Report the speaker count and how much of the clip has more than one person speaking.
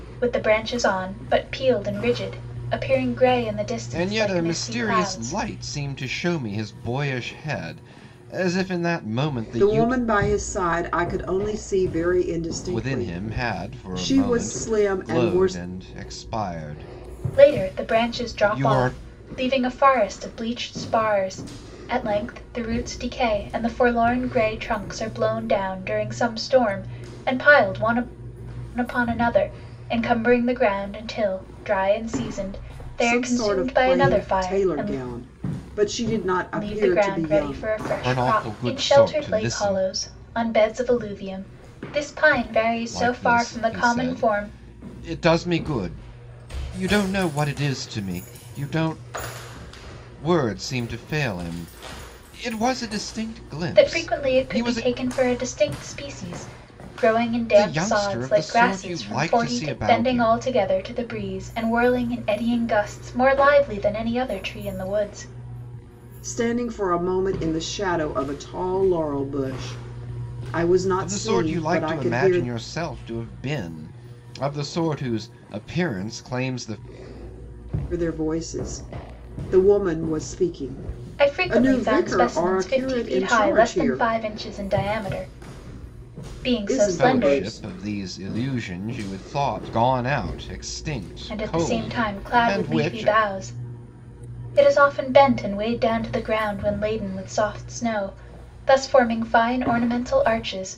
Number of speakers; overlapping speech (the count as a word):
three, about 24%